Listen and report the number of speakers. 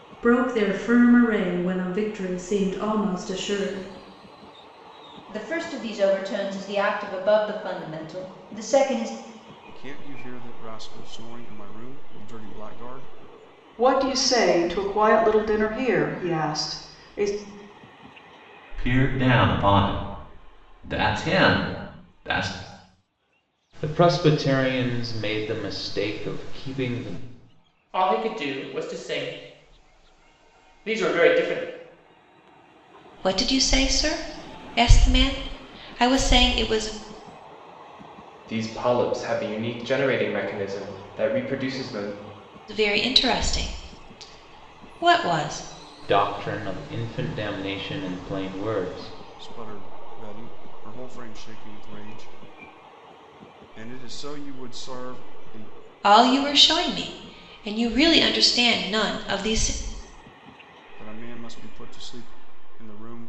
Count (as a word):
nine